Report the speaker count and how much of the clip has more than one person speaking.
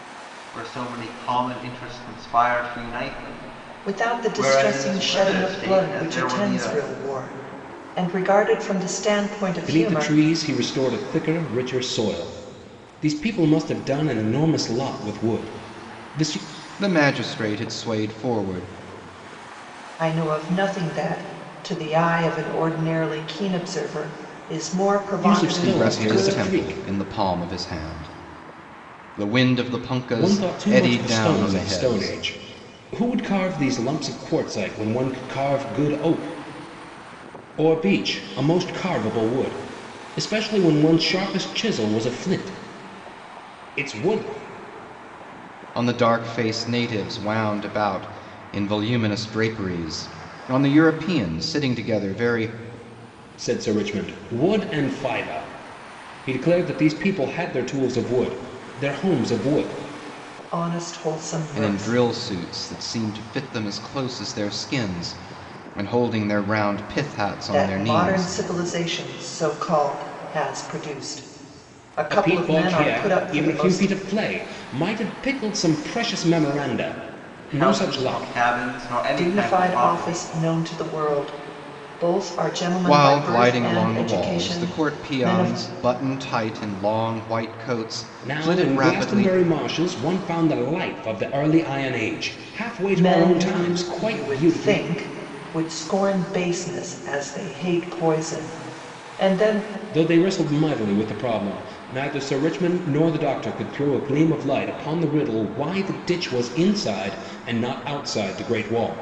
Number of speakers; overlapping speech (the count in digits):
4, about 17%